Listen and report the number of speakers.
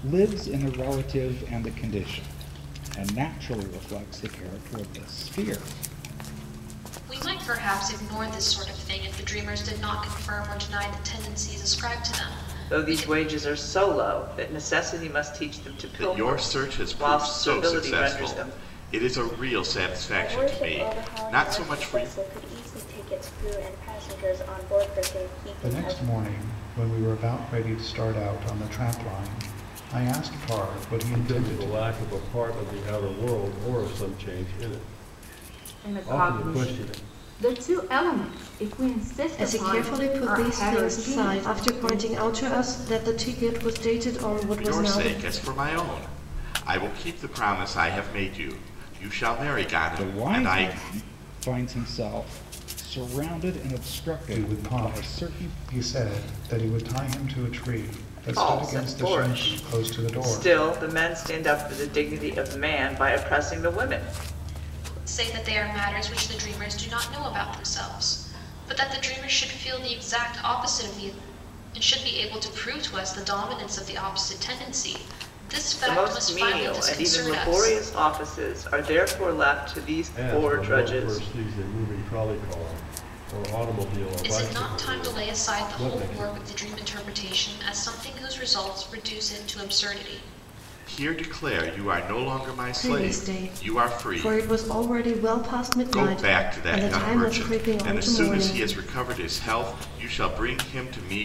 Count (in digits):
9